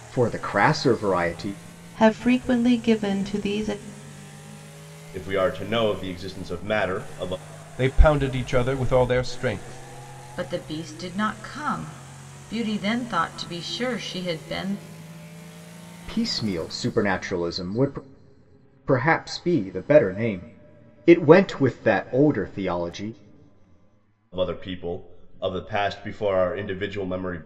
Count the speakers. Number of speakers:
five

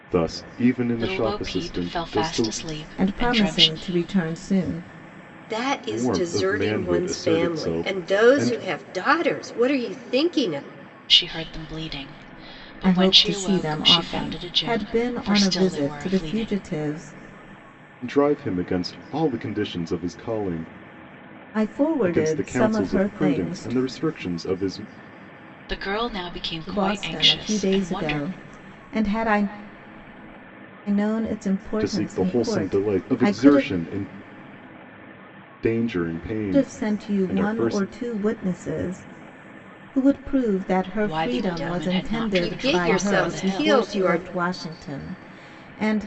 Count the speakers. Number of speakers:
four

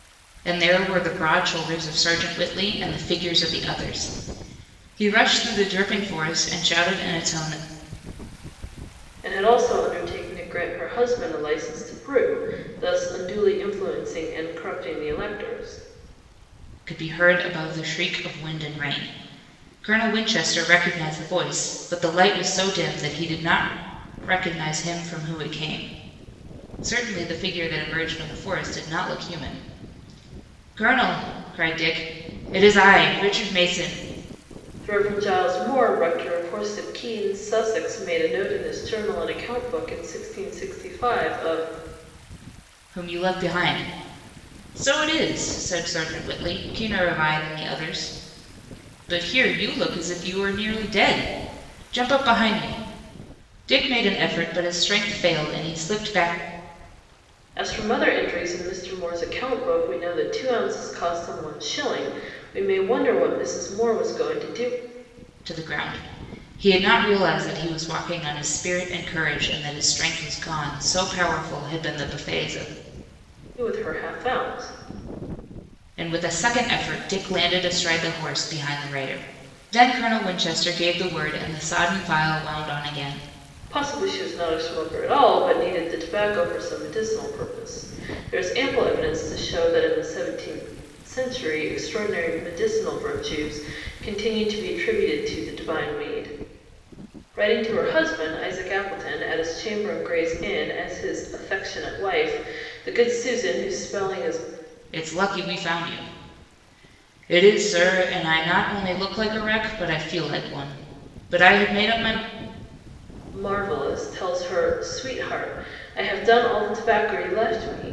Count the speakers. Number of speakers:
two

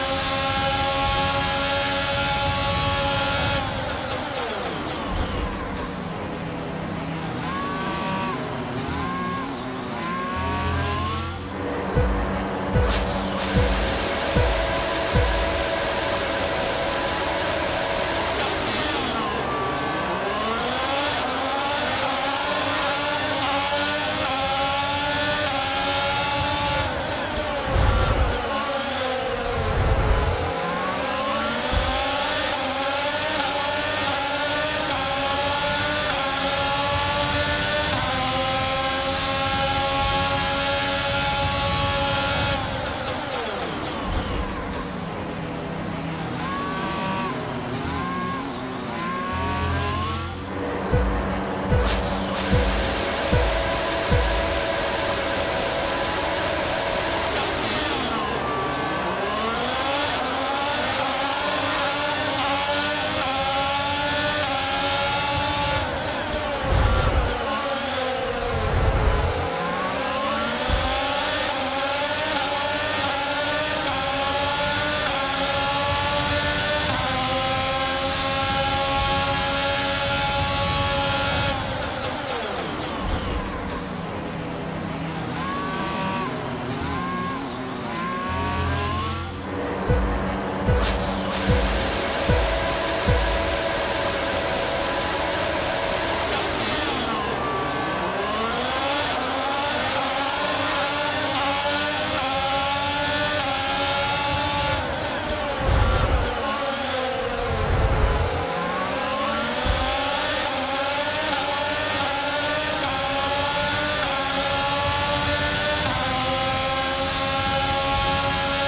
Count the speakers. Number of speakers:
zero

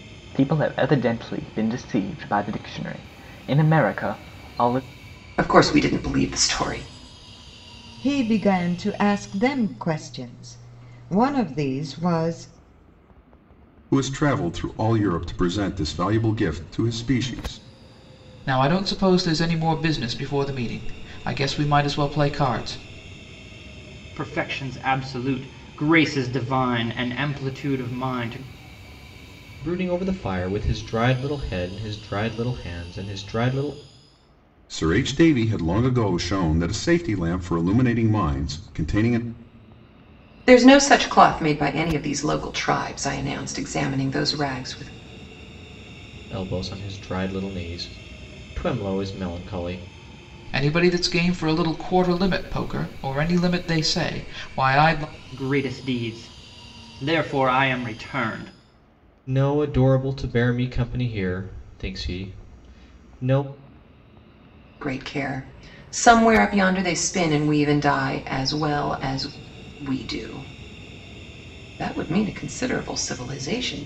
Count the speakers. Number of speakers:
seven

